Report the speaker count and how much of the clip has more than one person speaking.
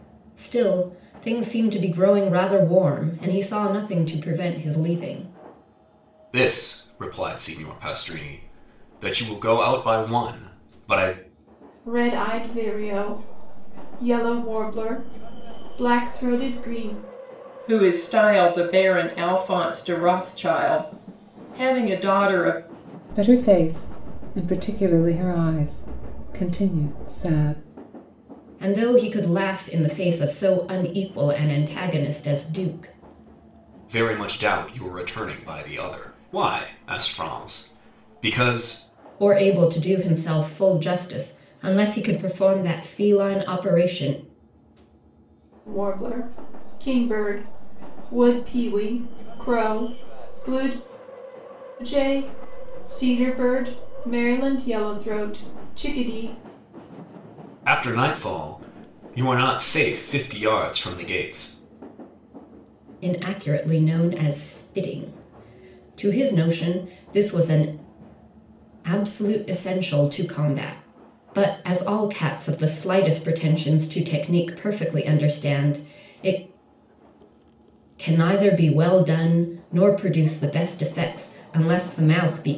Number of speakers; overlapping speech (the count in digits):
5, no overlap